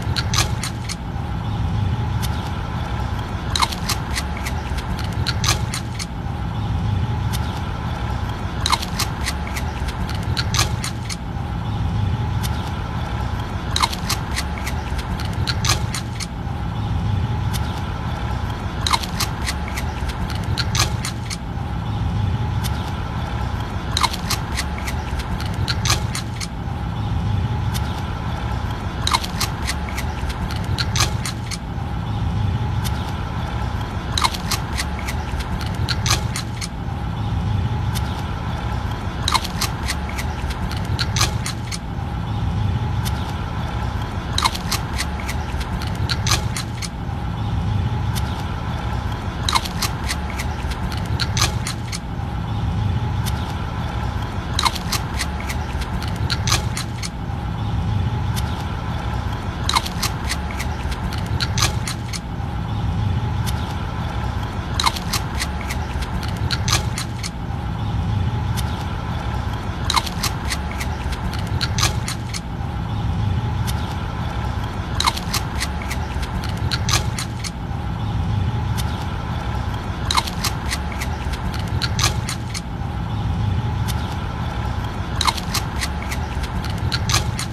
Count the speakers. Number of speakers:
0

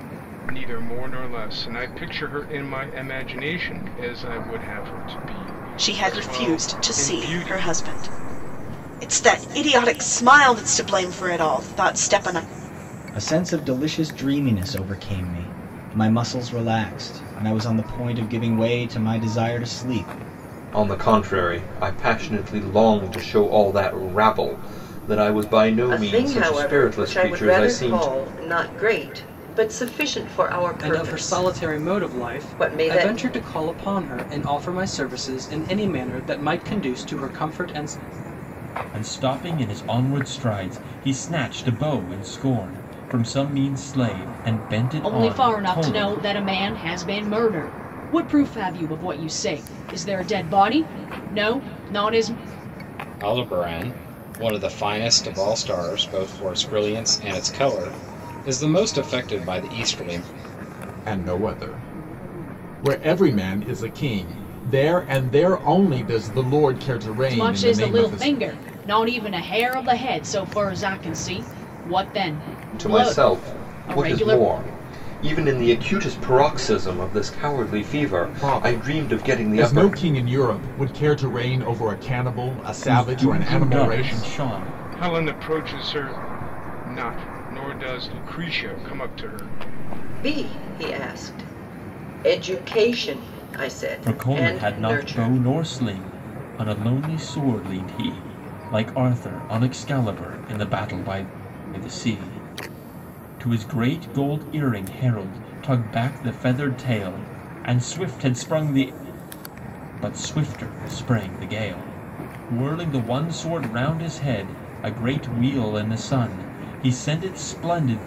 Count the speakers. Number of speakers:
10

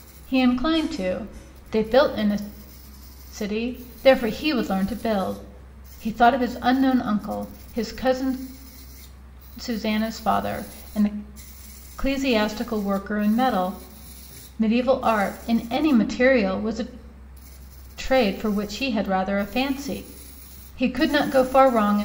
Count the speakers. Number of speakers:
1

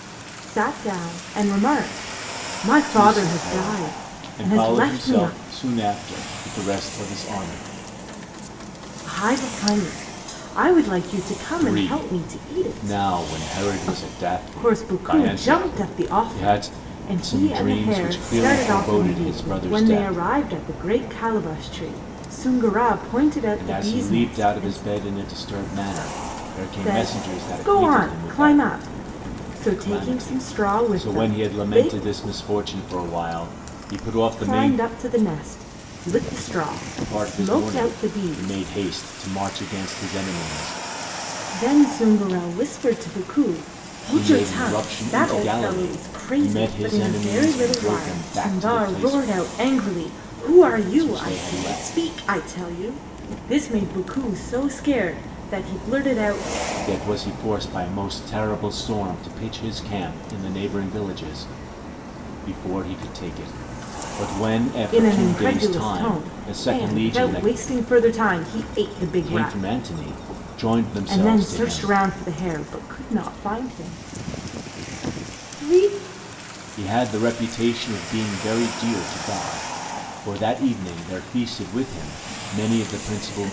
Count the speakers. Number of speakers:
2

